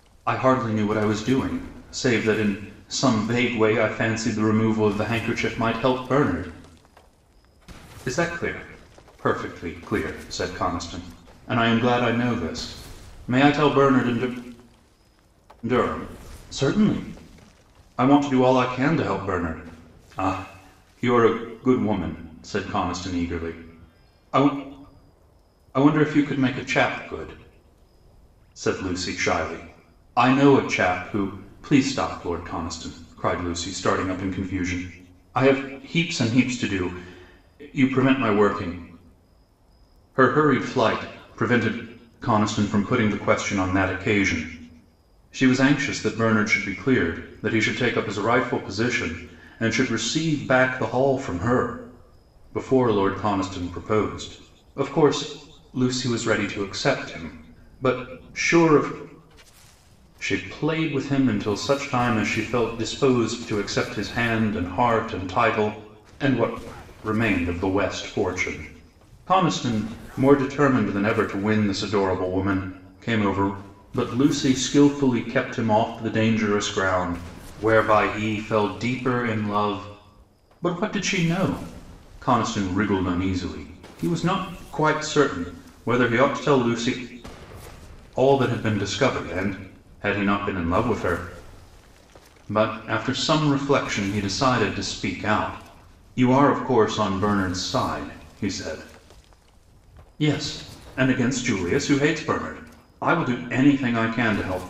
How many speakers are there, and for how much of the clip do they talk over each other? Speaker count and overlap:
1, no overlap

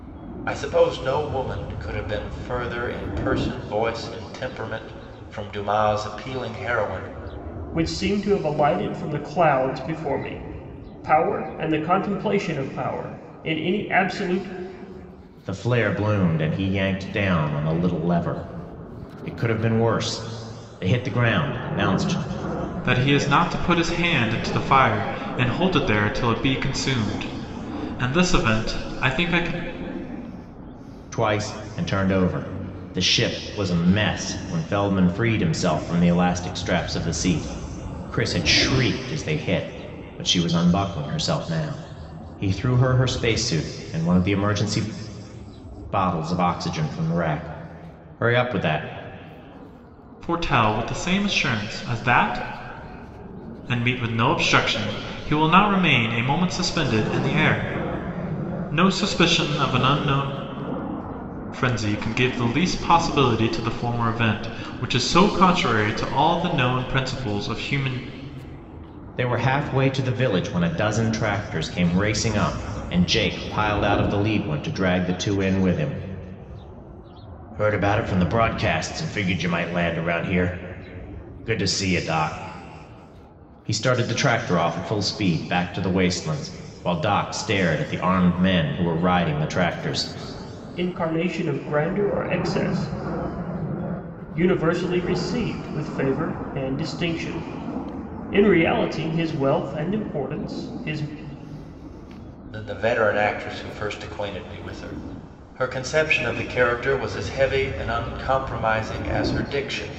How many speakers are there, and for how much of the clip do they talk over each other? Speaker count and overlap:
4, no overlap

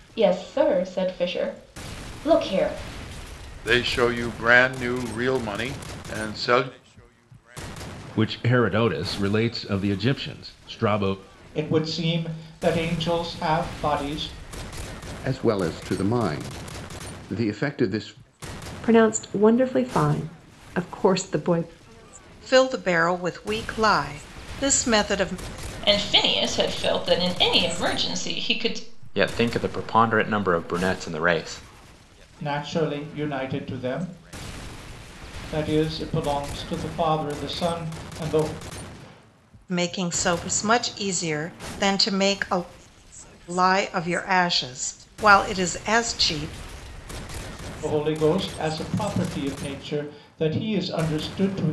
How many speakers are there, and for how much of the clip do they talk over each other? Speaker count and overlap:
9, no overlap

